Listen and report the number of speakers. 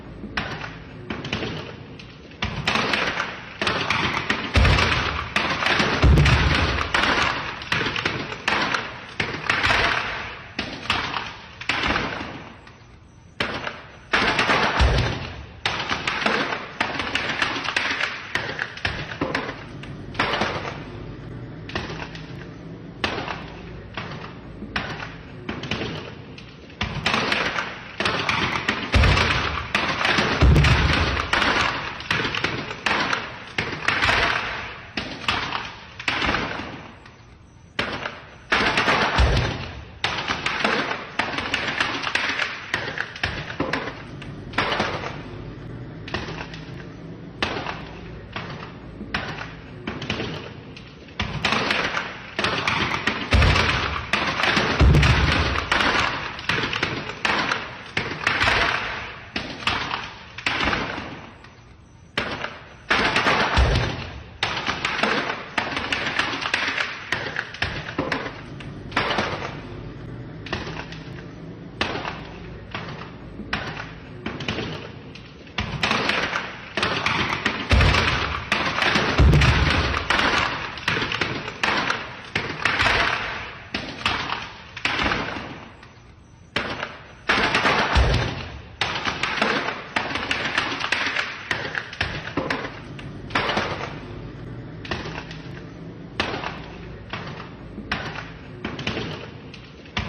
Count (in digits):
0